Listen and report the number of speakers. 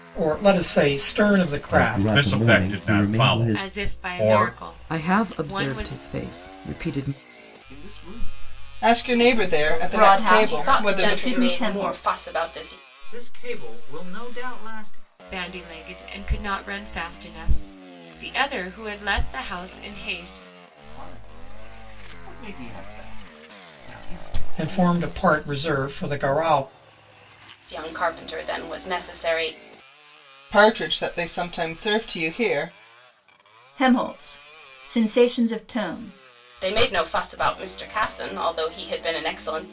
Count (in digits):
10